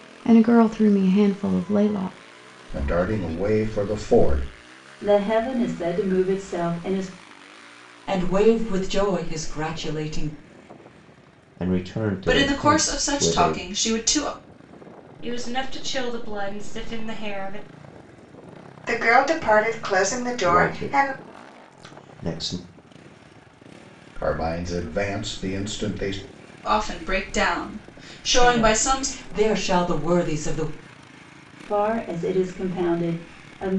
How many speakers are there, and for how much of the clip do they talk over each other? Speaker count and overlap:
8, about 9%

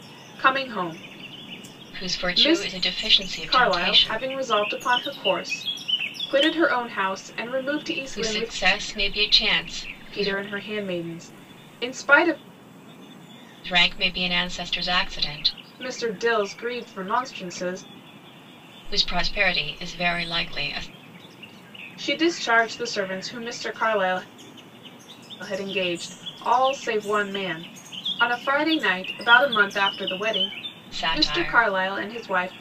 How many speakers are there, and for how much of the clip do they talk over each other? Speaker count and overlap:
2, about 10%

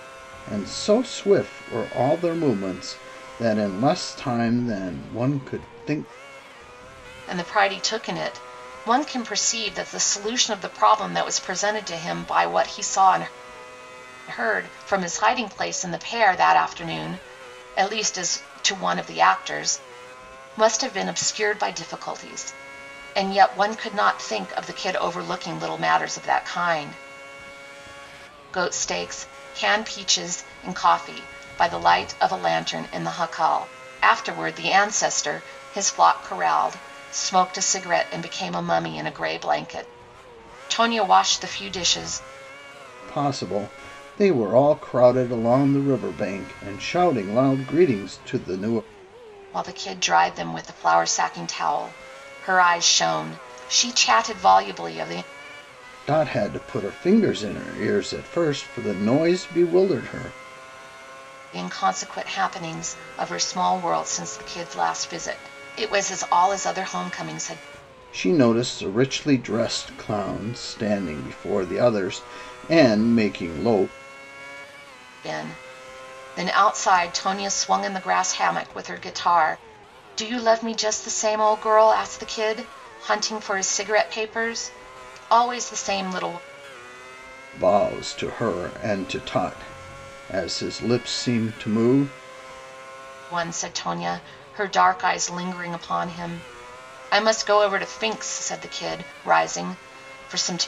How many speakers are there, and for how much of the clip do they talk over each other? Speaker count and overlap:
2, no overlap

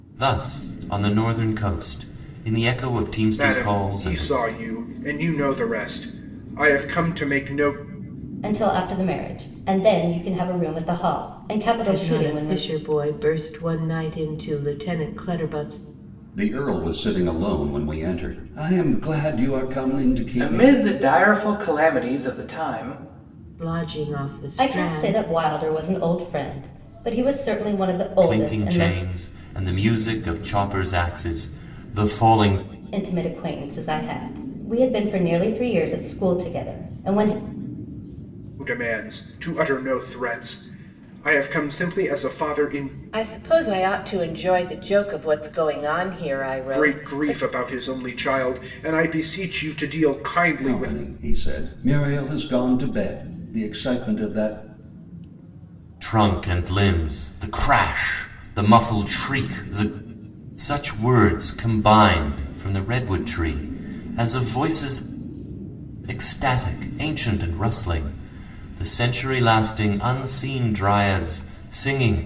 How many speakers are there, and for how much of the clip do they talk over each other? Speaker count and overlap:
6, about 7%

